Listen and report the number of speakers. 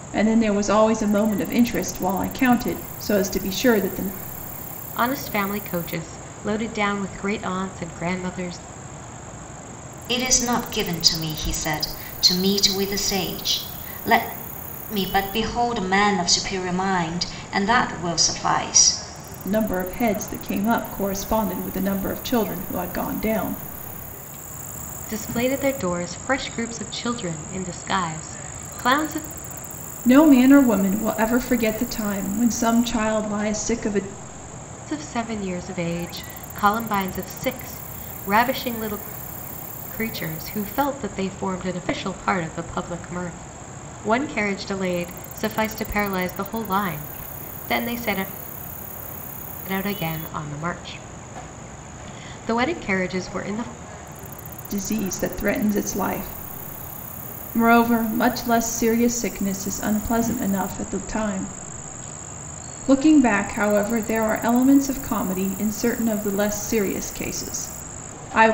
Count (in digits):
3